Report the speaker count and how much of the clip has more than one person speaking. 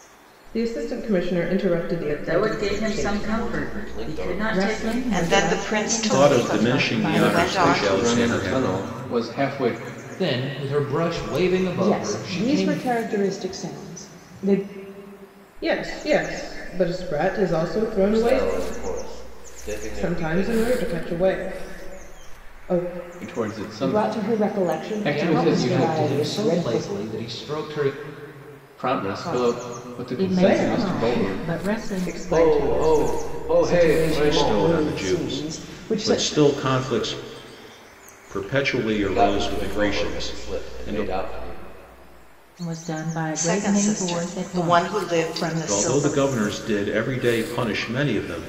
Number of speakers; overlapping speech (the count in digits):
9, about 49%